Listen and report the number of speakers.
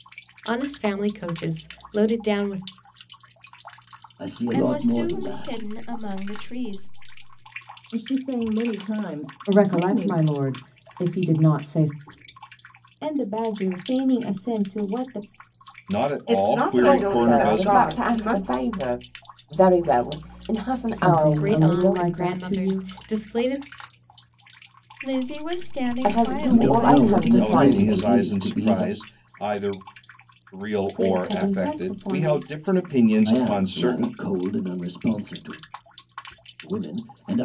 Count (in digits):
9